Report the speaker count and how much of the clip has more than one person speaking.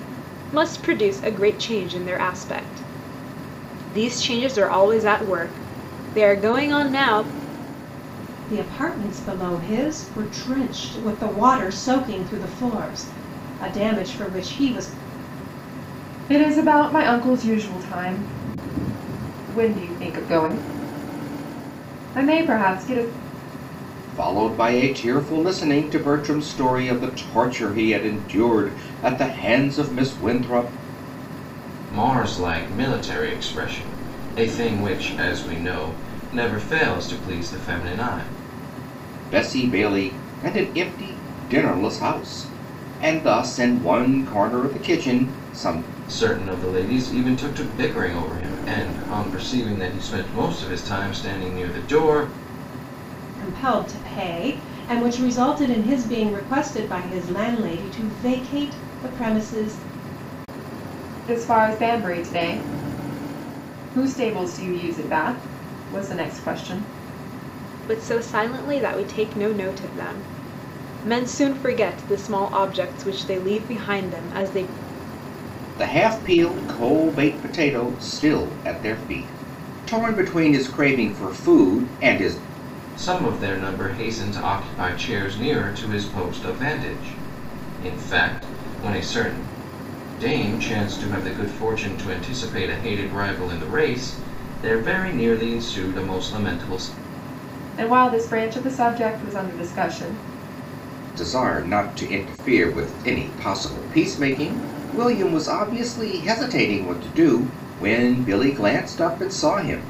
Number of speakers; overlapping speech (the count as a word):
five, no overlap